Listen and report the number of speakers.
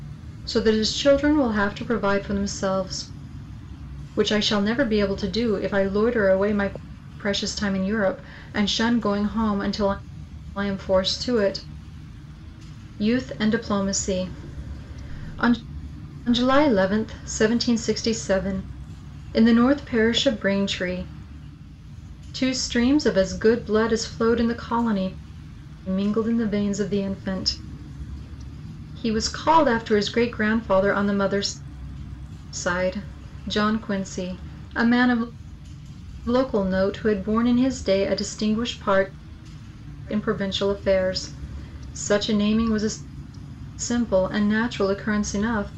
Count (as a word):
one